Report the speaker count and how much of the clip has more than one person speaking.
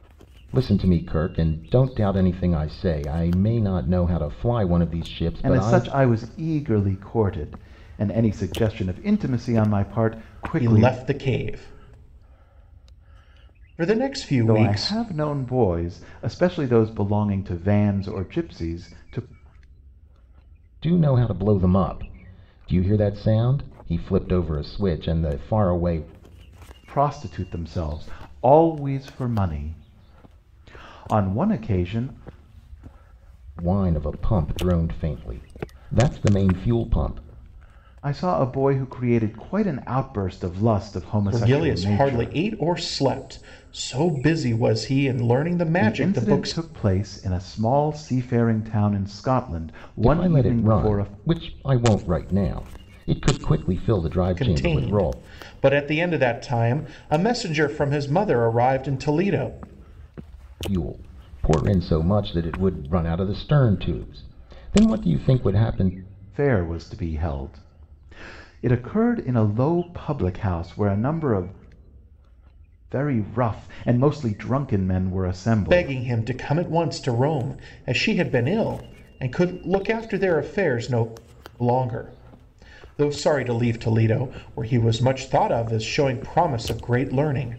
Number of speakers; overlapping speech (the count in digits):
3, about 7%